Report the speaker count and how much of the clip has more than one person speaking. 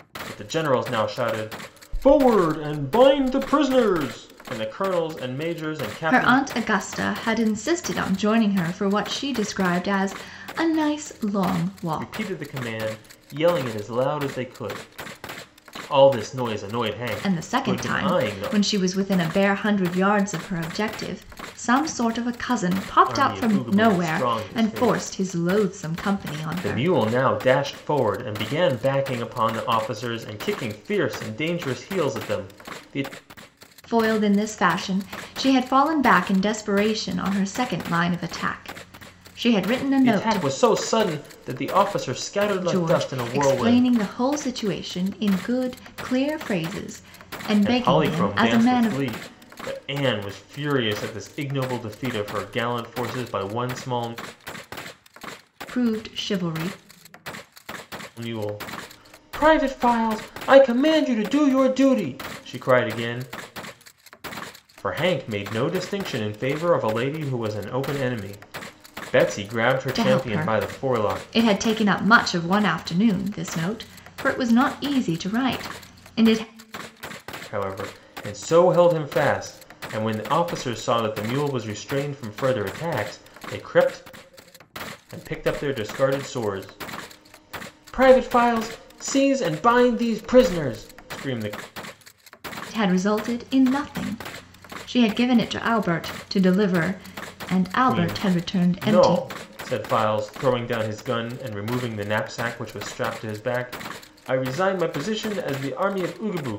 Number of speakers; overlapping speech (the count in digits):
2, about 10%